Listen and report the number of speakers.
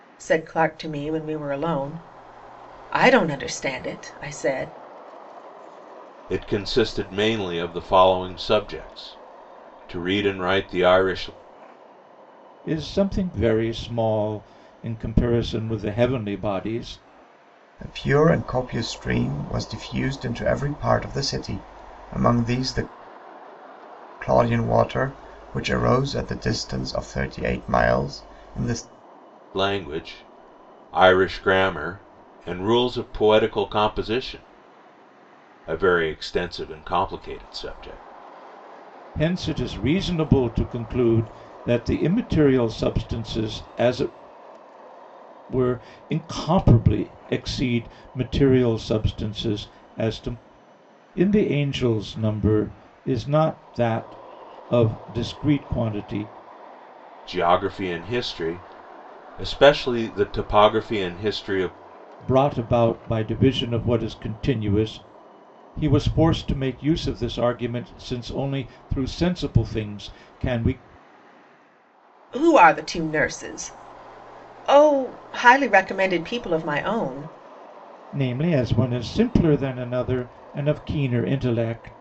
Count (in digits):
4